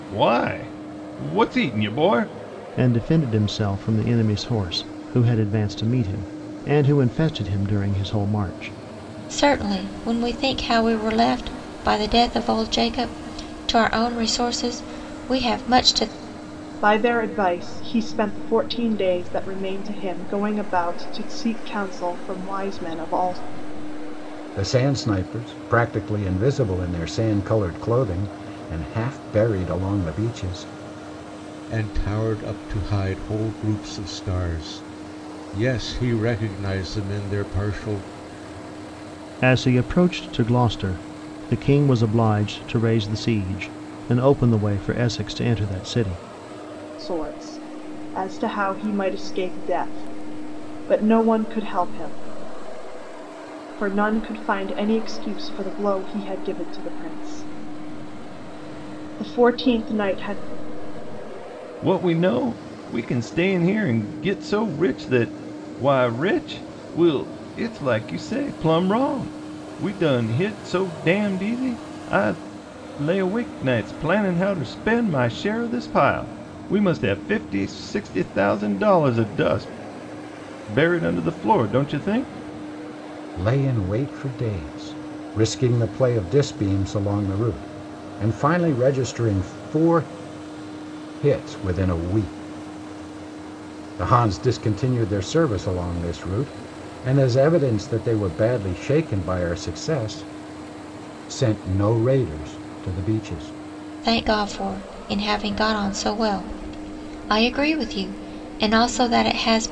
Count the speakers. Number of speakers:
6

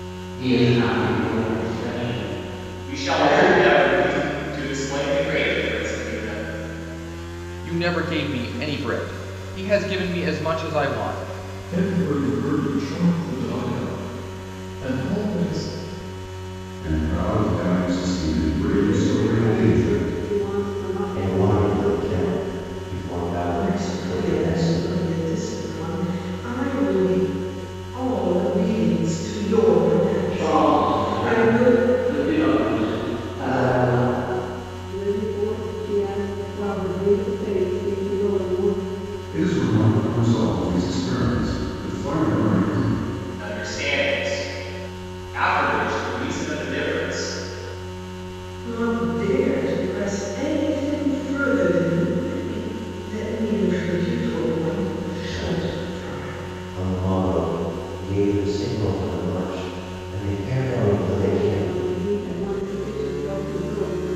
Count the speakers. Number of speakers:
8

